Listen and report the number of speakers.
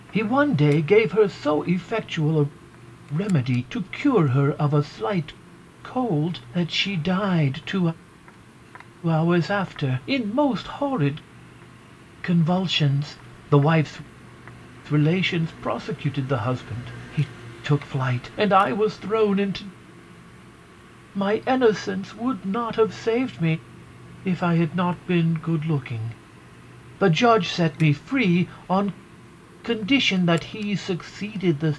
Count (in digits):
1